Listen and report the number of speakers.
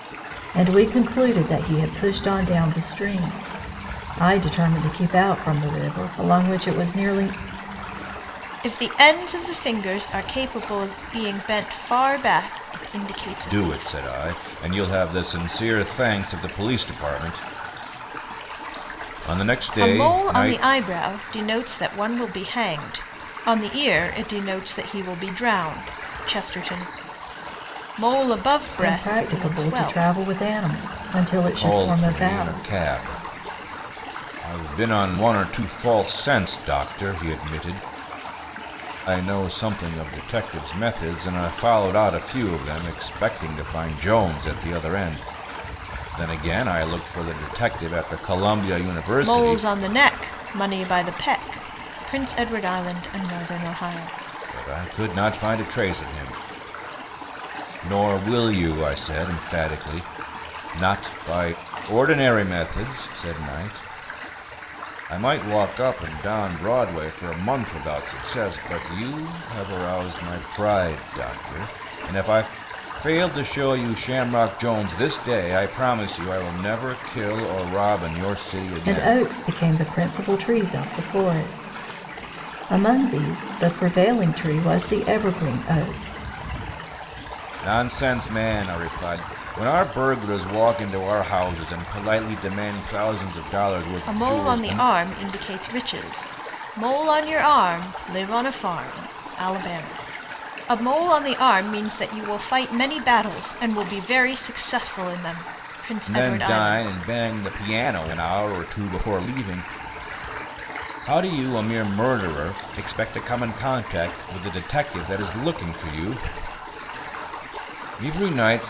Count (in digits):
3